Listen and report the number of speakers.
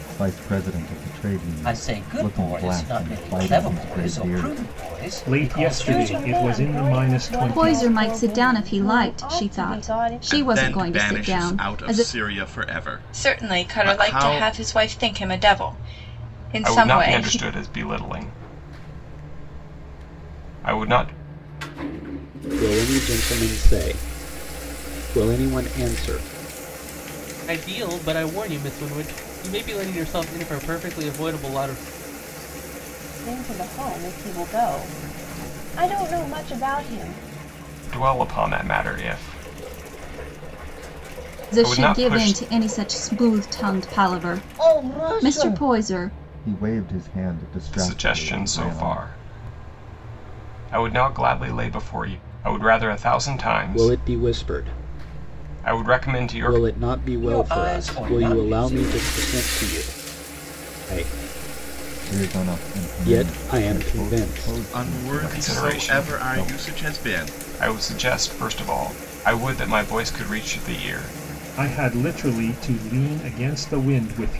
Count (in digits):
10